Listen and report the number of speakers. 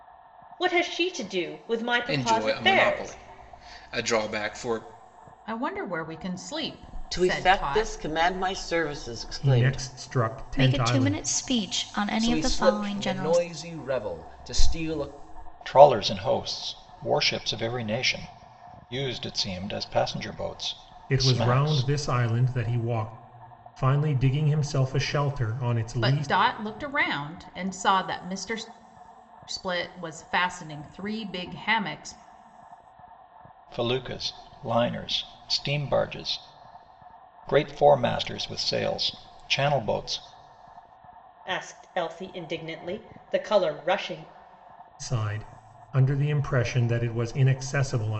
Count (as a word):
eight